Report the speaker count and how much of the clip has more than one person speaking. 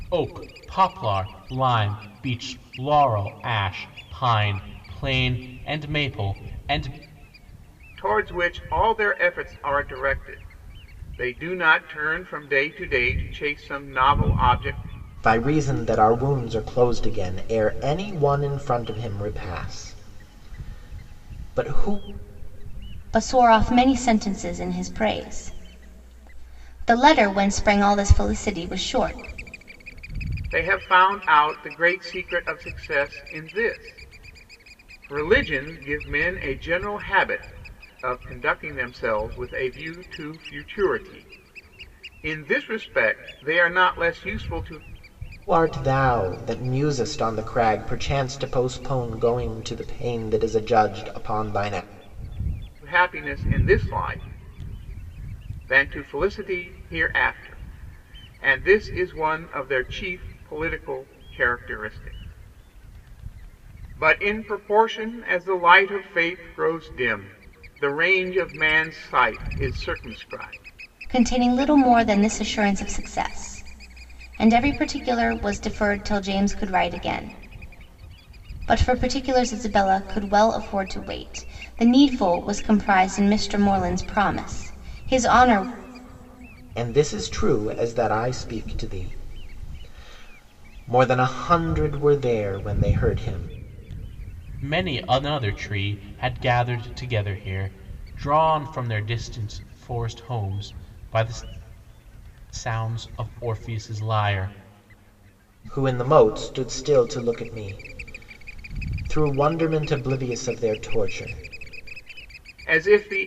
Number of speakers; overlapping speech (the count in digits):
4, no overlap